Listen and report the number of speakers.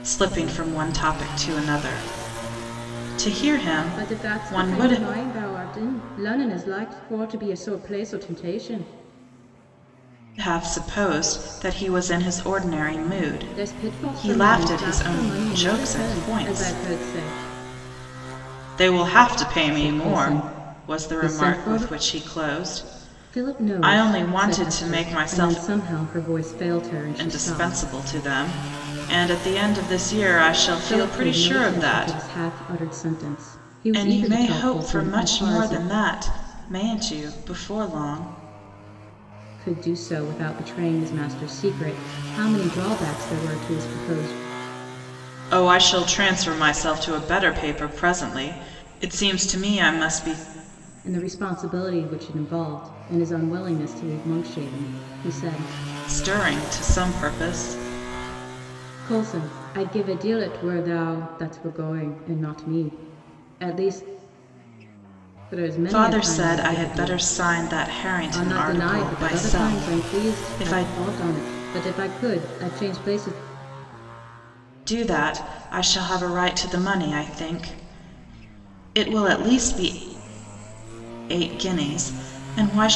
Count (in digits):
2